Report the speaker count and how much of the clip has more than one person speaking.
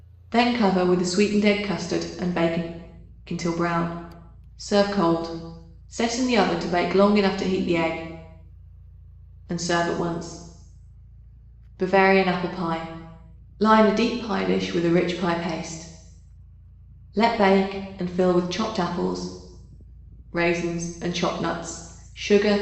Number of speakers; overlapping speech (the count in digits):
1, no overlap